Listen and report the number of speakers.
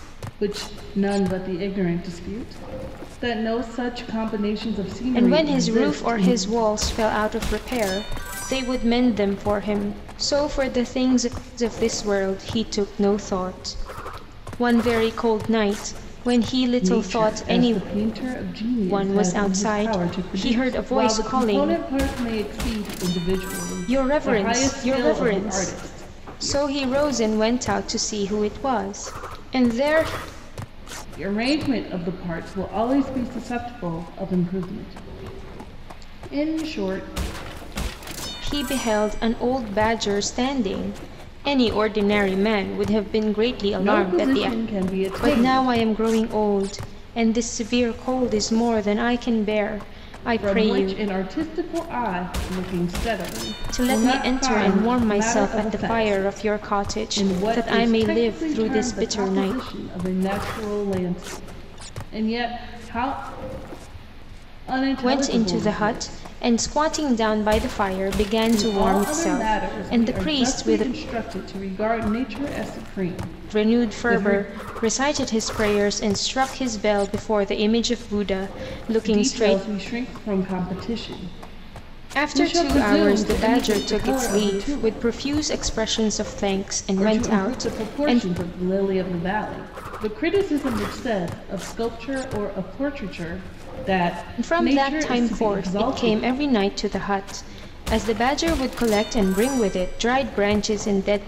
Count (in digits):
2